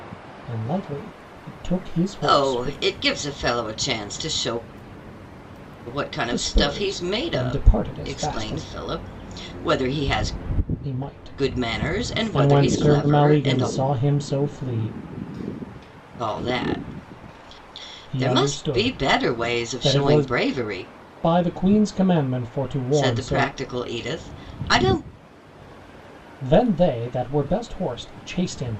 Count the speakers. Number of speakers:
two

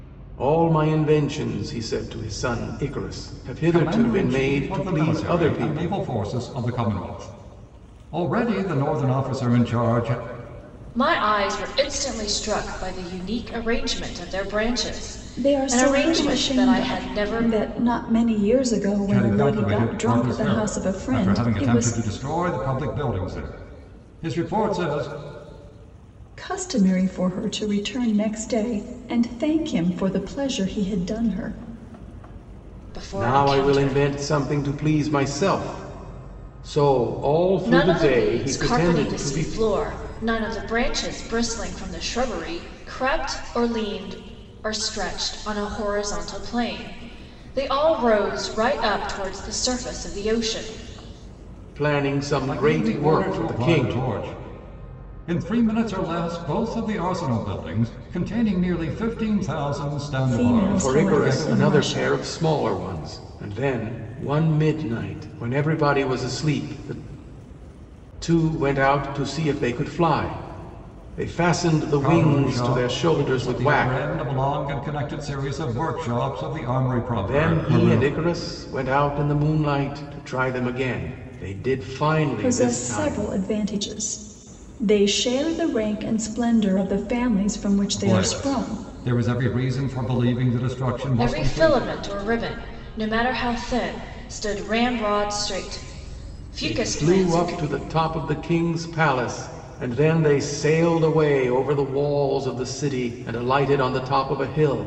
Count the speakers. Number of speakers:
four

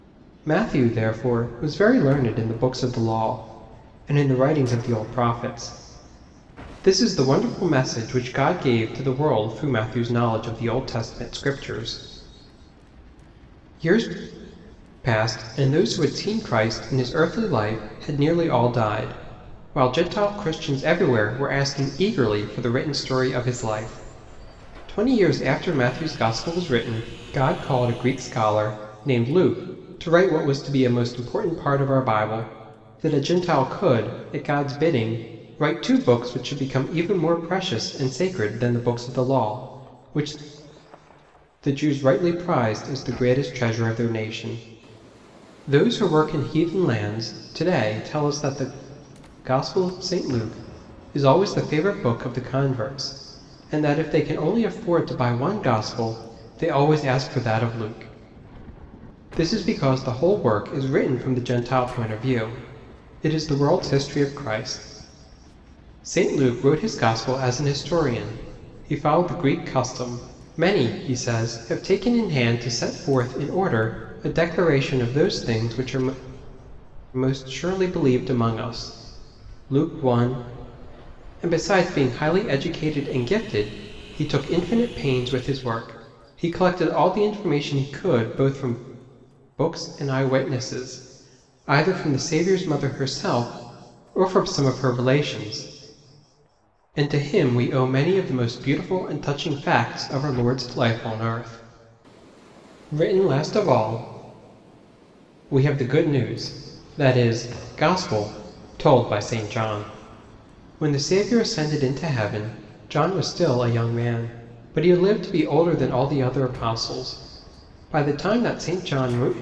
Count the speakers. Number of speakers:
one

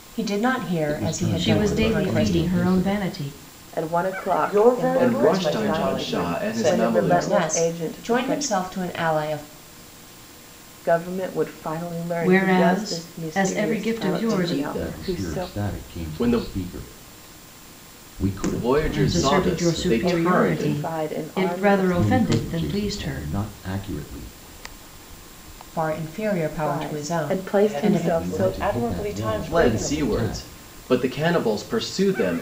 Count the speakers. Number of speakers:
six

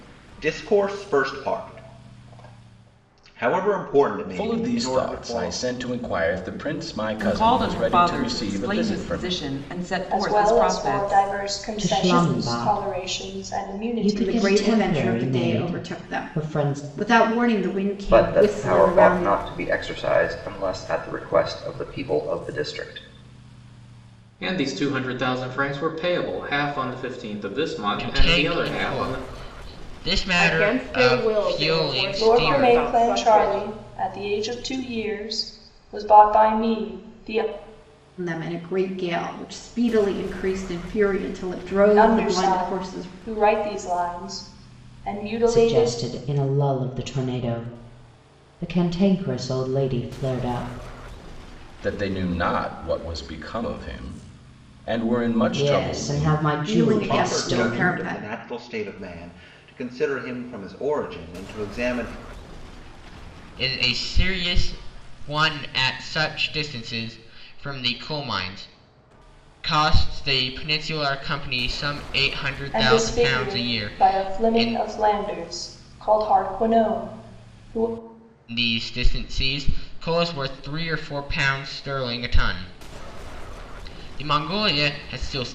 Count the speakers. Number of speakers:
ten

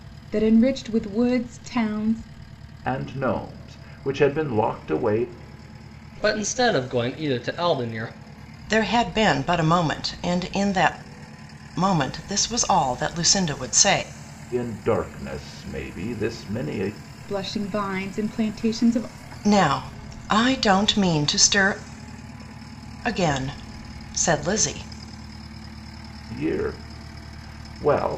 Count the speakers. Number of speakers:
four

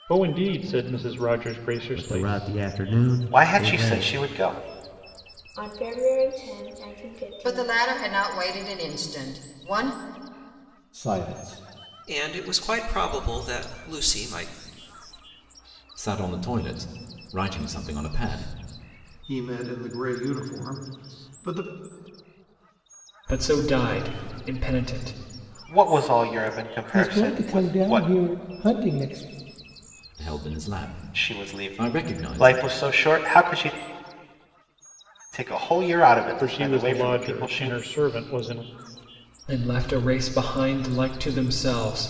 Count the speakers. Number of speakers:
ten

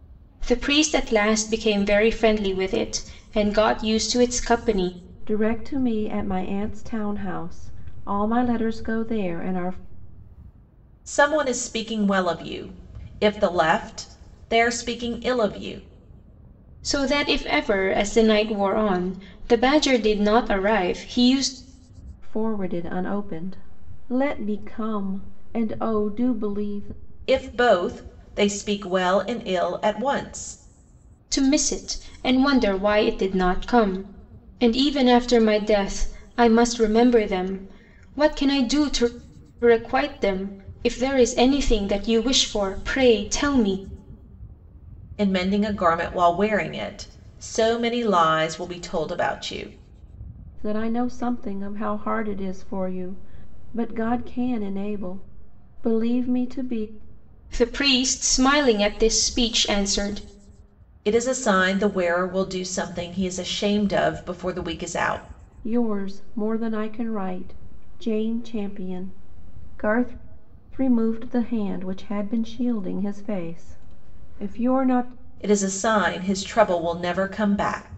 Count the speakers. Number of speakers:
three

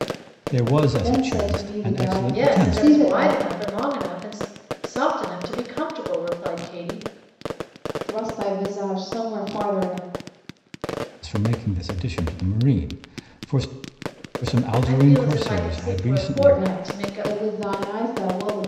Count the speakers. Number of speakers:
three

